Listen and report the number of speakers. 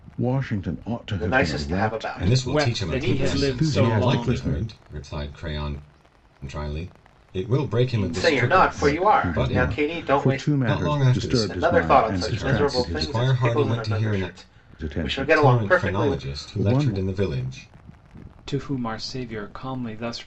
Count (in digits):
4